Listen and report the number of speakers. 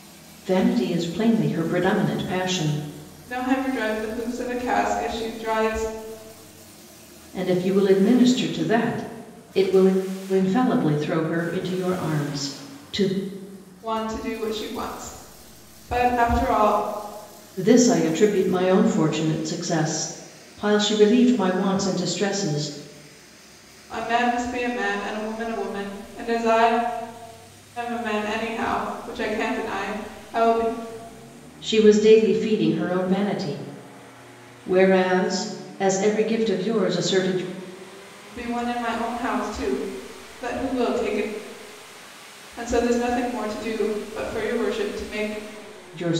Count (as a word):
two